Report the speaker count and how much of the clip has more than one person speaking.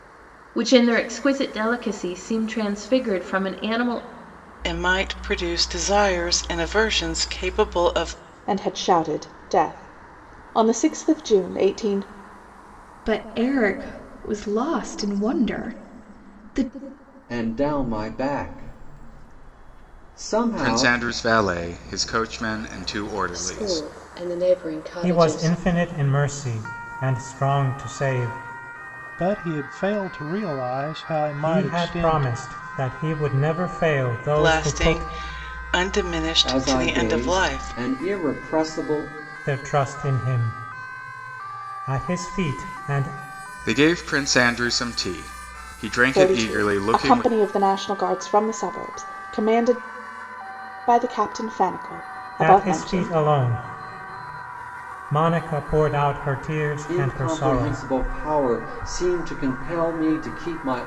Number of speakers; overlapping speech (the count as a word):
nine, about 13%